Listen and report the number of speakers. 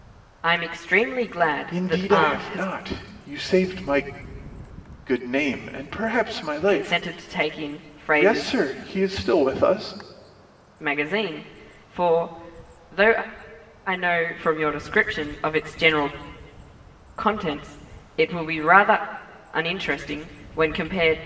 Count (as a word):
two